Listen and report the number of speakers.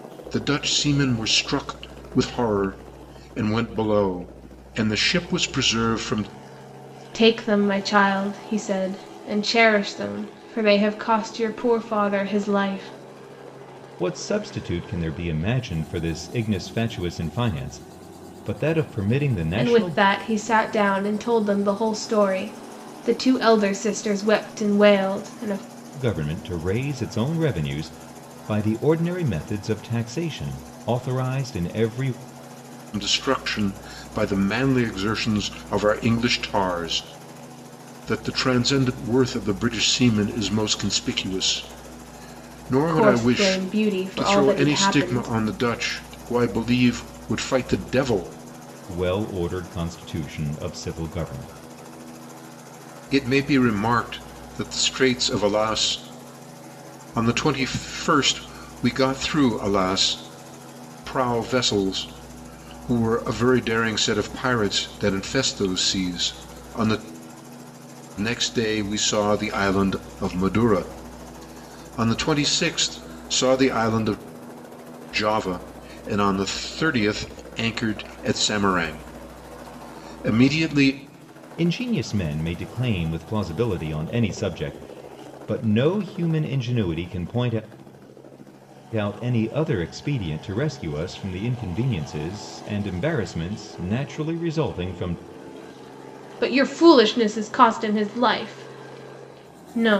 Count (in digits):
3